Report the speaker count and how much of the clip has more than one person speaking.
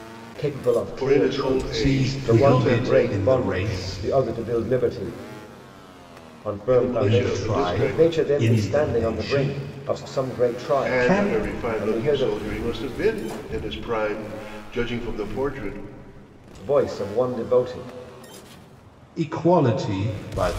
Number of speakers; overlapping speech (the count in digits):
3, about 43%